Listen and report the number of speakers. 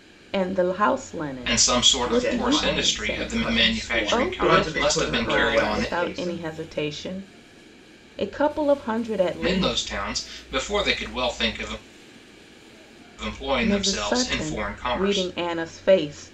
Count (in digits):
3